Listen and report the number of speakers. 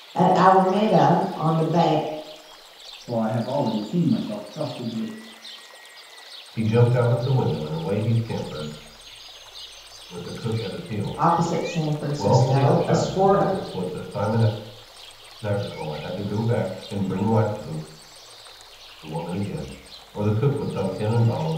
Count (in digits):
3